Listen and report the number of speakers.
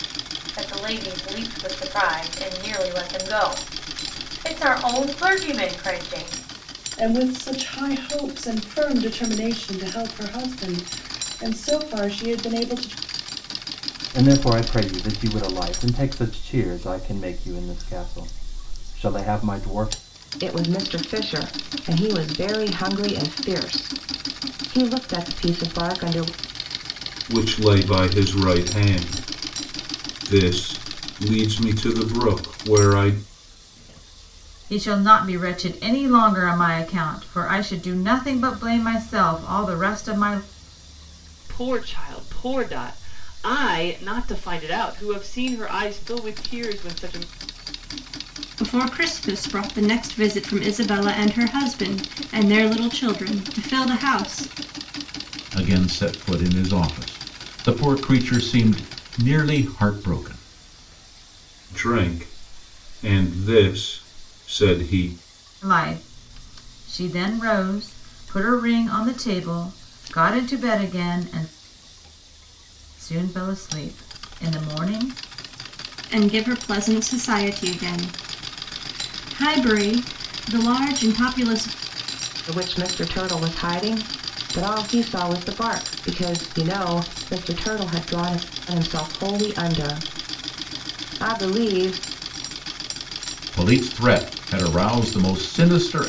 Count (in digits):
9